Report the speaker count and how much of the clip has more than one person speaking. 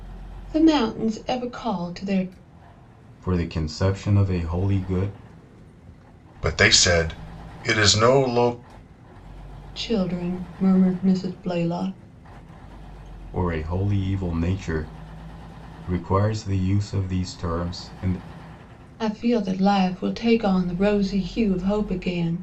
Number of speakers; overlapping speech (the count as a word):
three, no overlap